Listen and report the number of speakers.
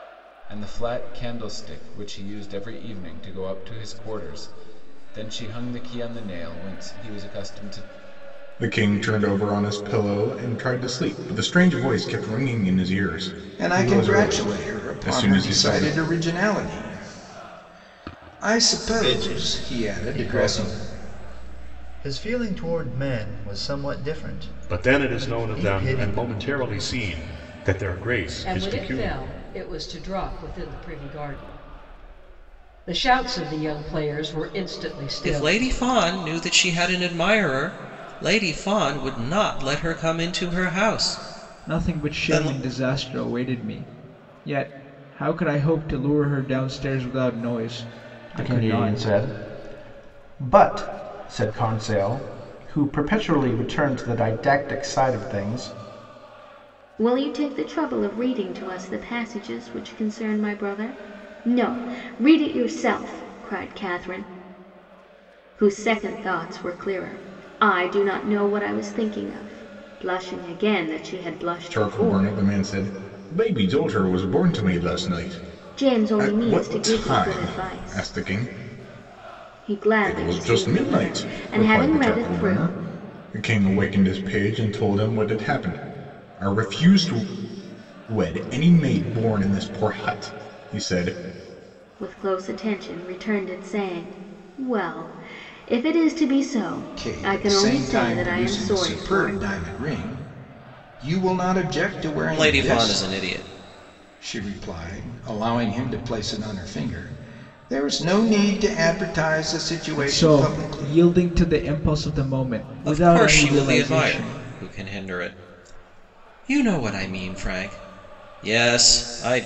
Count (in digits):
10